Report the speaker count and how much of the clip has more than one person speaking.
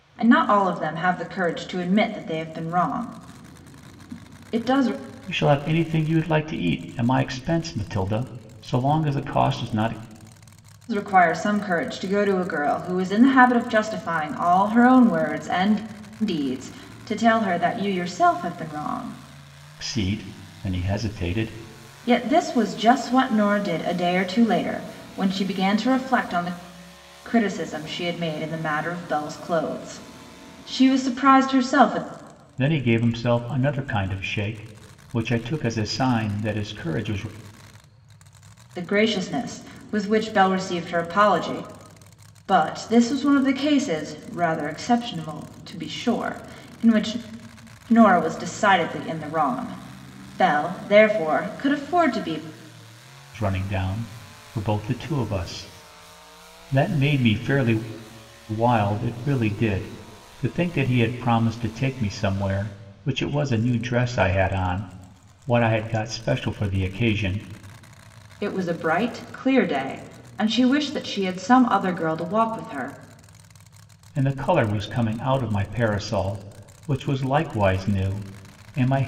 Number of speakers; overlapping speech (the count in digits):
2, no overlap